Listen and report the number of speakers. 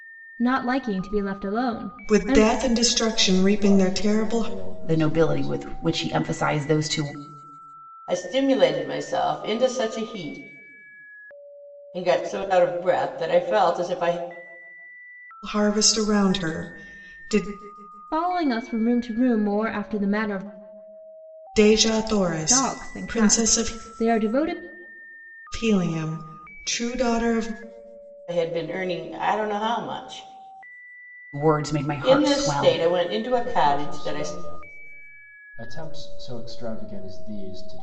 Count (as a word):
five